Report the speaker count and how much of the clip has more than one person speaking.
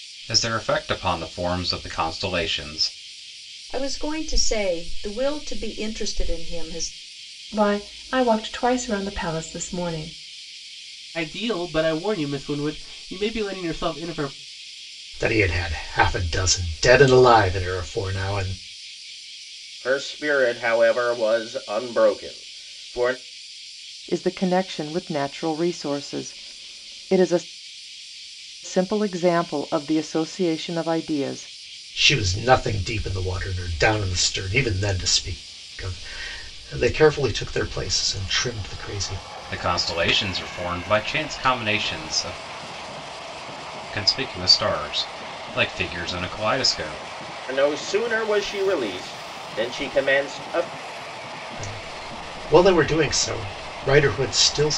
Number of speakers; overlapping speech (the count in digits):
7, no overlap